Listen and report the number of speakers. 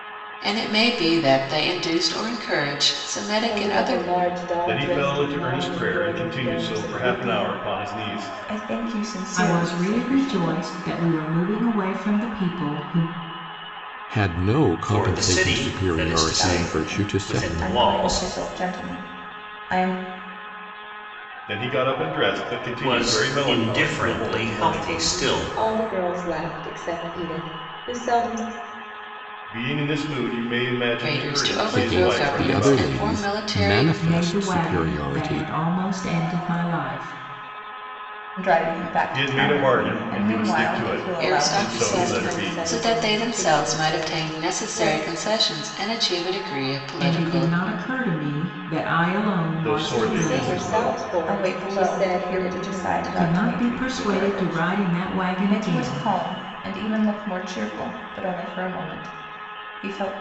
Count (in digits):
7